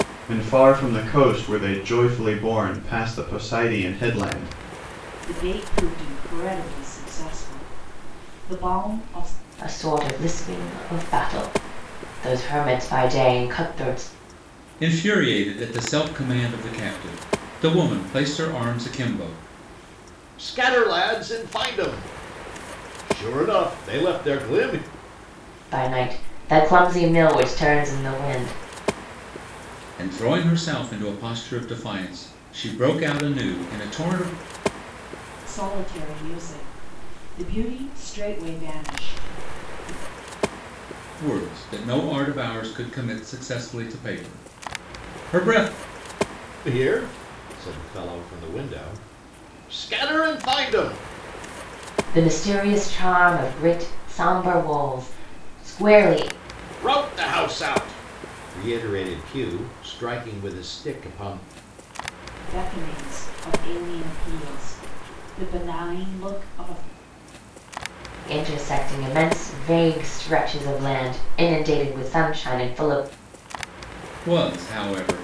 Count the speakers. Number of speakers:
5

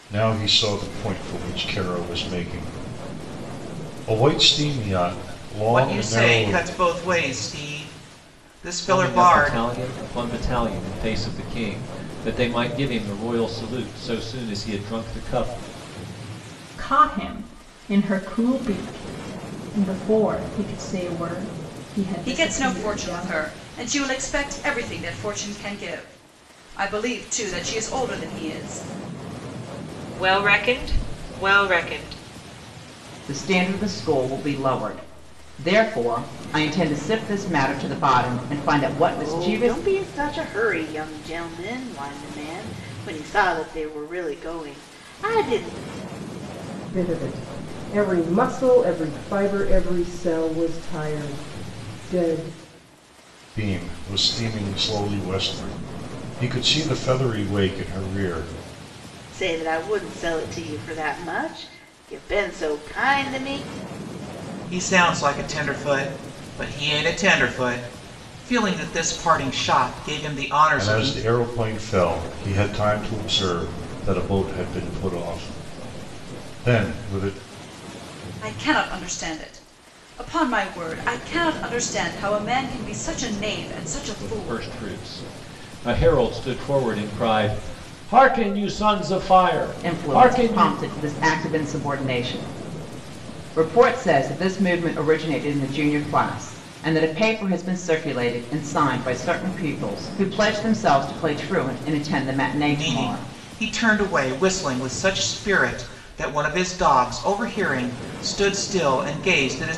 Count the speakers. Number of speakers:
9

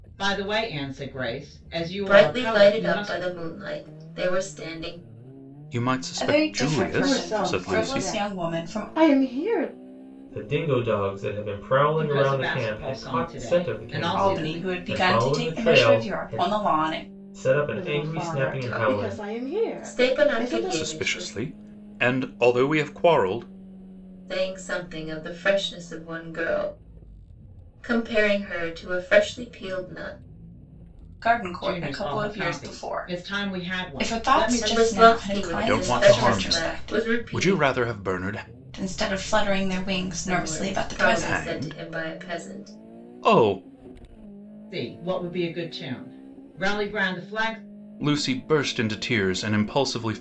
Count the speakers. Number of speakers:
6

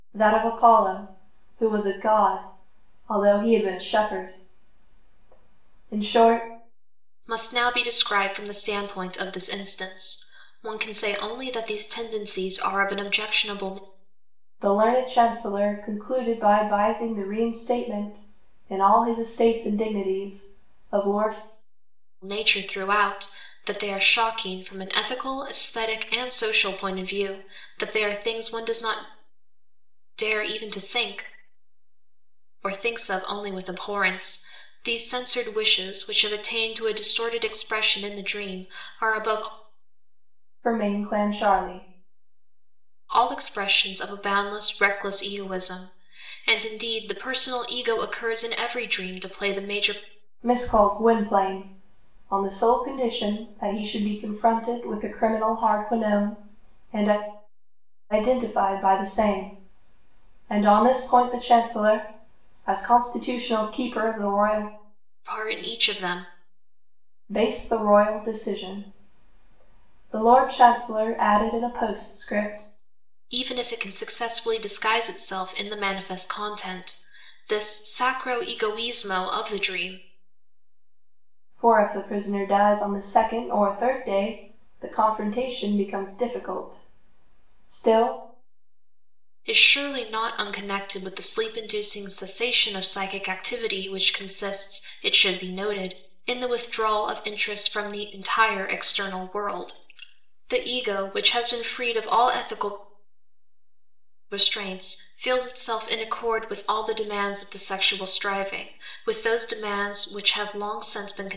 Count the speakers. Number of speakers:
2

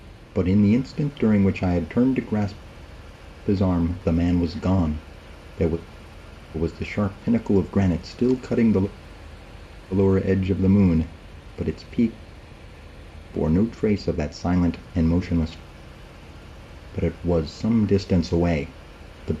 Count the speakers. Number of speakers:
1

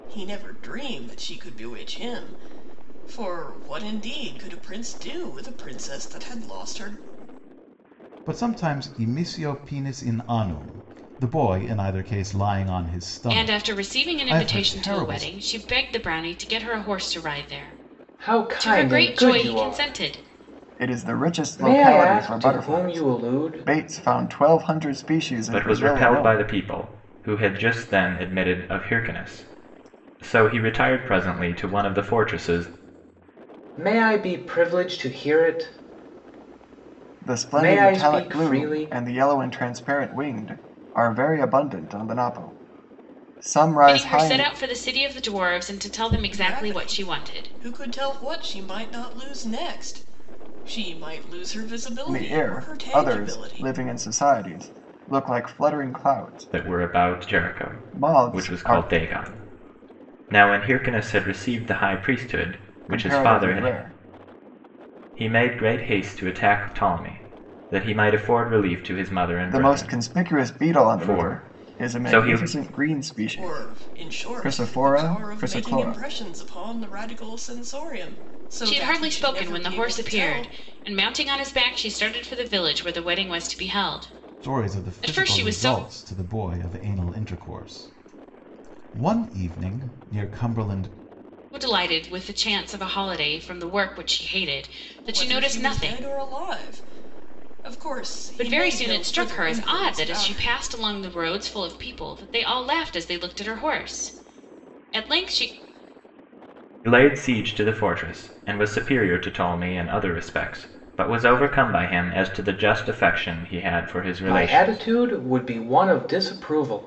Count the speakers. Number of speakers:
6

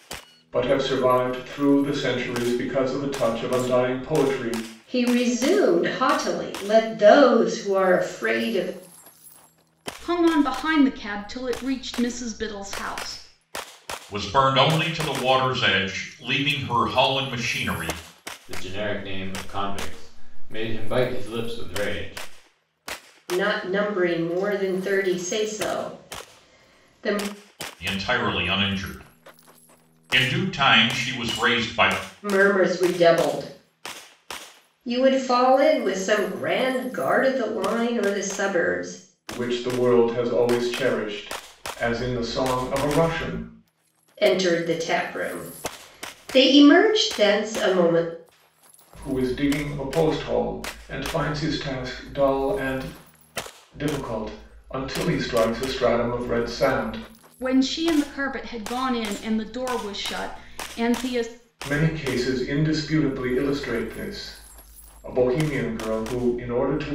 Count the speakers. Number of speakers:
5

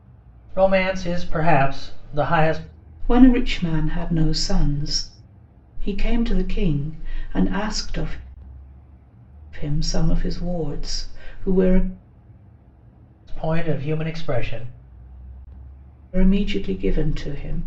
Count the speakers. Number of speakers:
2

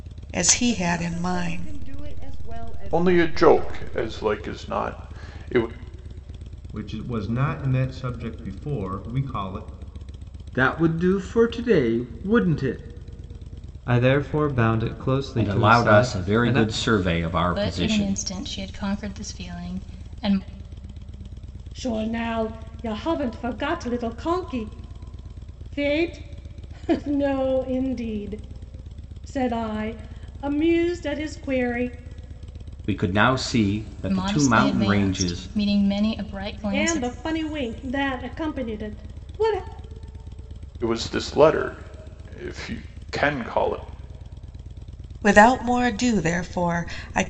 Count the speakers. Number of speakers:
9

